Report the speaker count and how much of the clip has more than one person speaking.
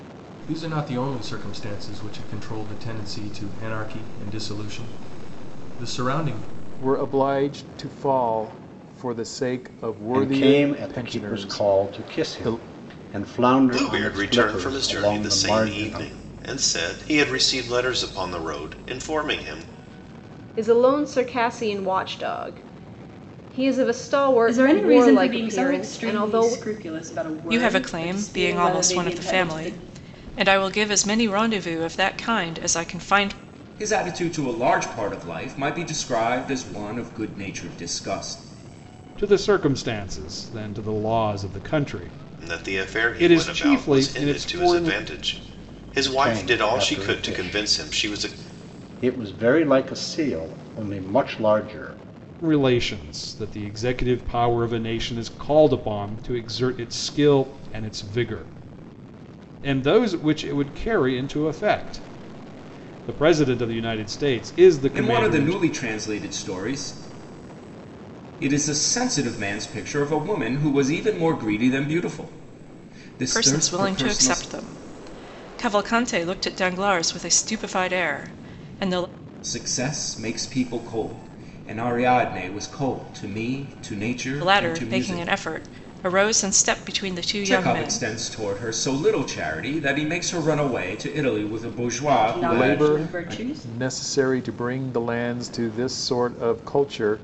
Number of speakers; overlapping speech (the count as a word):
nine, about 20%